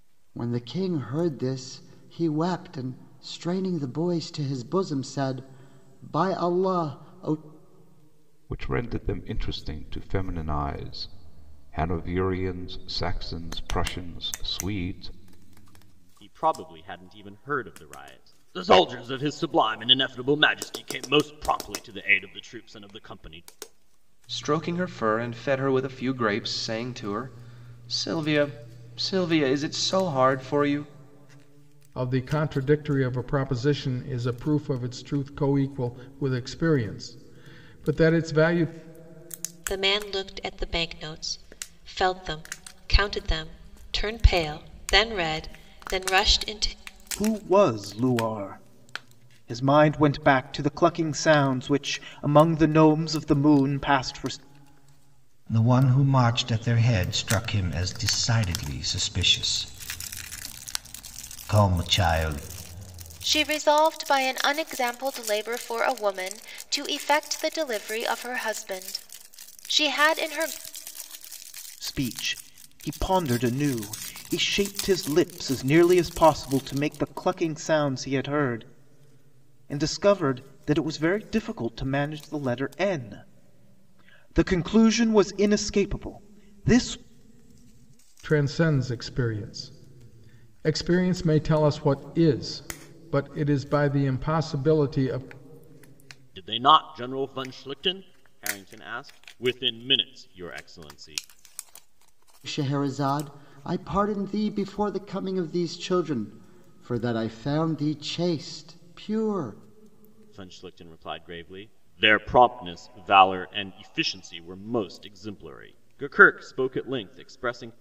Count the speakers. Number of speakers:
nine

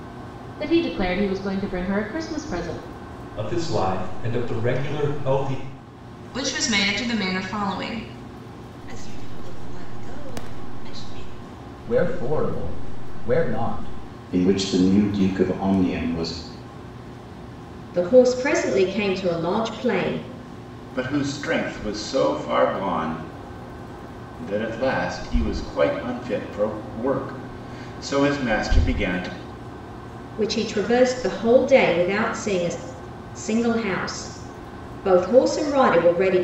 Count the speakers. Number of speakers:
eight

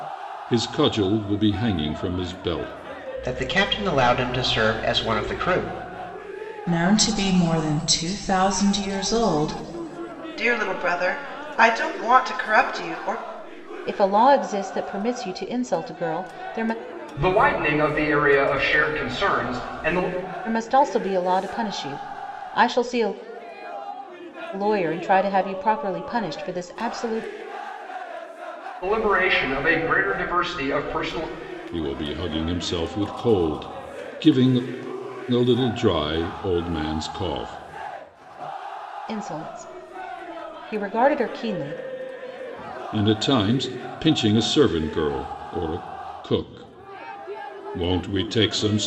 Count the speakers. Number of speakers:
six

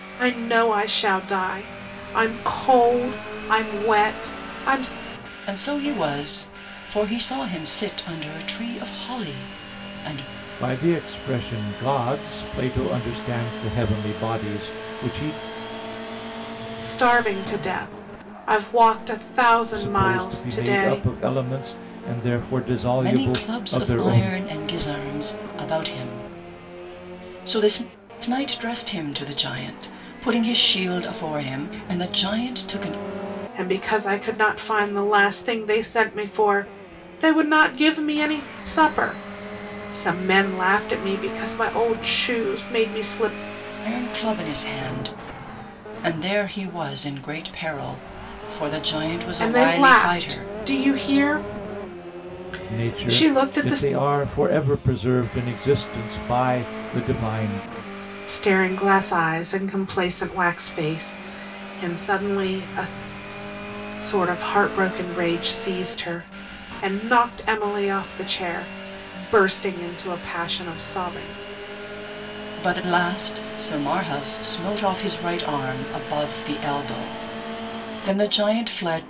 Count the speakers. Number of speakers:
three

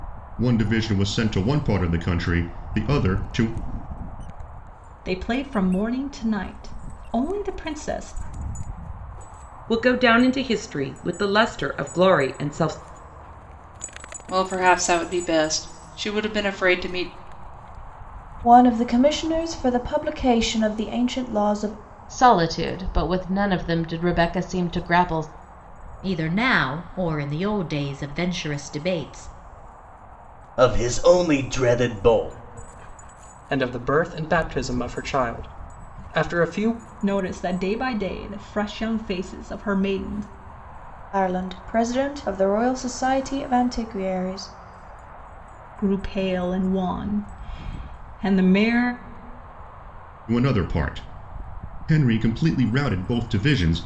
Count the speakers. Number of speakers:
nine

